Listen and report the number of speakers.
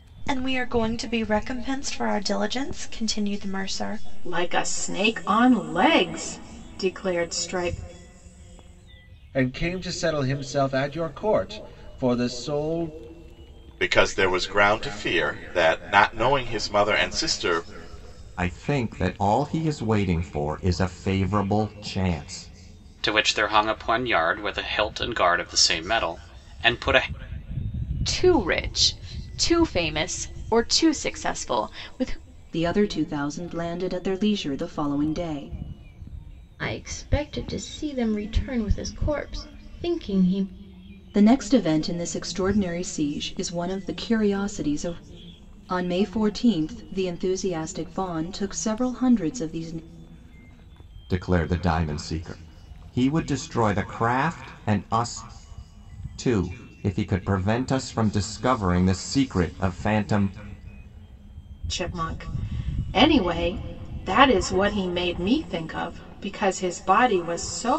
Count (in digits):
9